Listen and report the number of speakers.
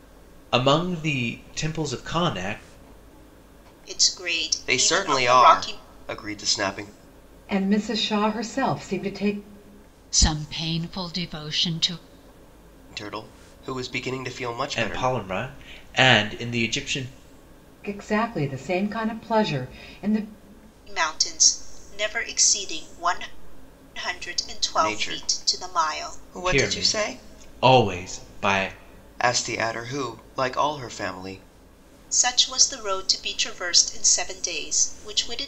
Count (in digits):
5